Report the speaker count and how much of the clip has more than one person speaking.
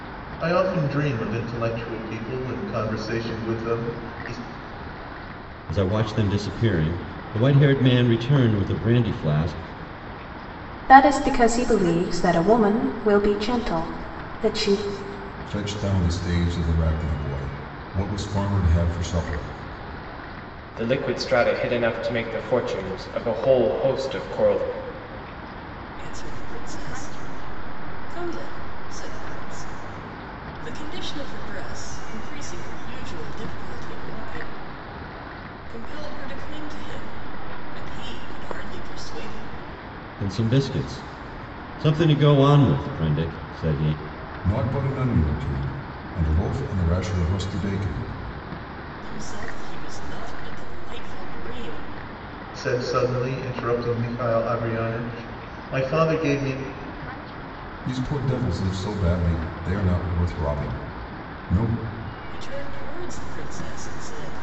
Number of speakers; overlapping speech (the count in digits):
6, no overlap